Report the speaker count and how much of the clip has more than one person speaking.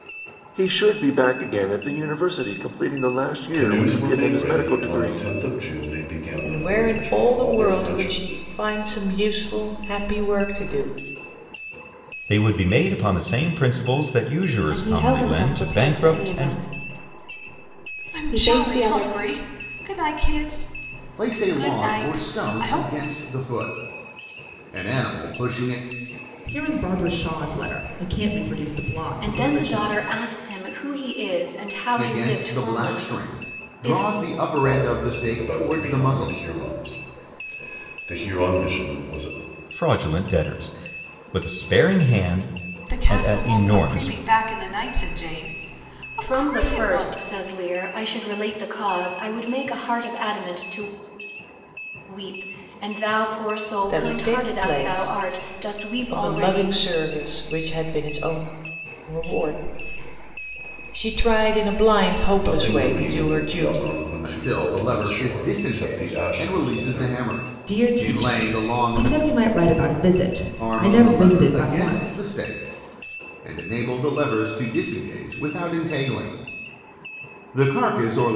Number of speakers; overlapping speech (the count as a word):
nine, about 33%